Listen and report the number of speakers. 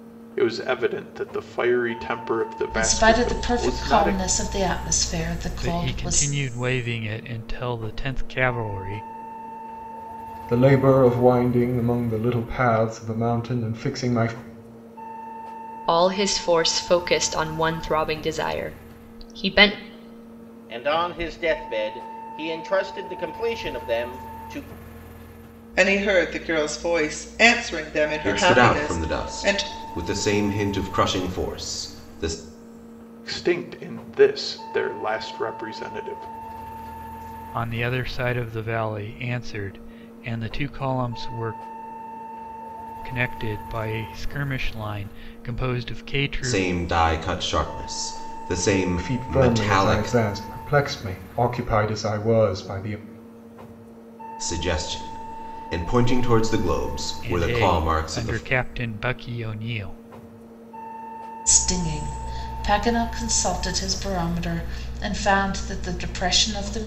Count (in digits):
8